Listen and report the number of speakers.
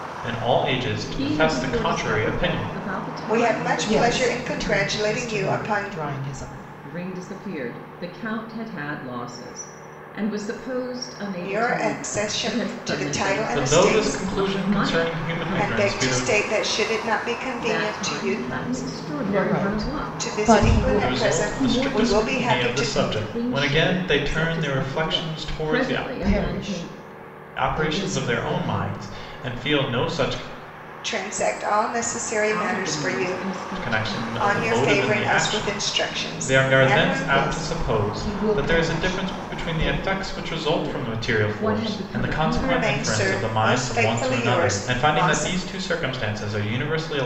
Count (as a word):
four